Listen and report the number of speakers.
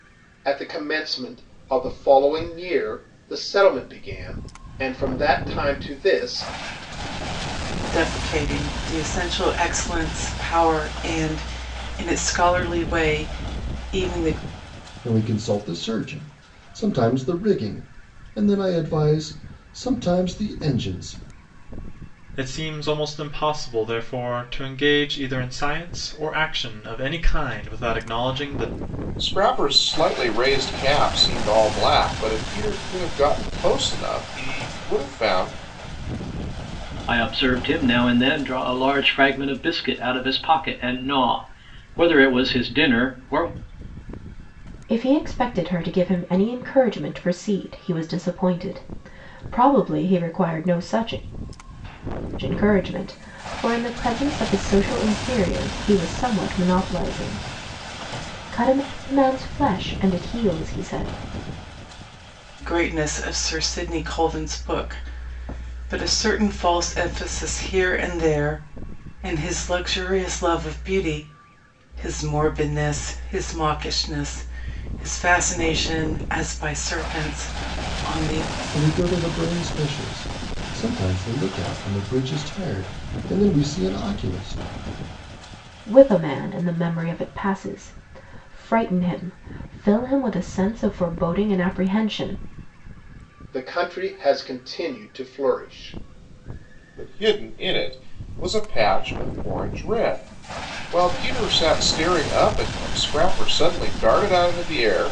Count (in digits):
7